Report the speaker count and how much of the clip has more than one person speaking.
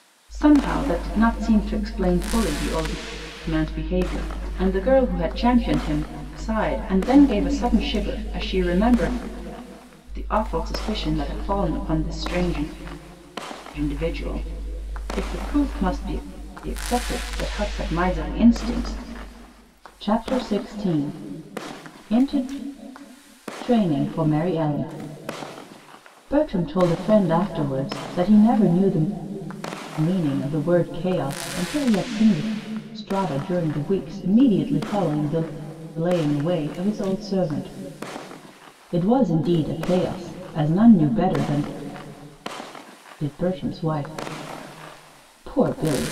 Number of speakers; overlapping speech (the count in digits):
1, no overlap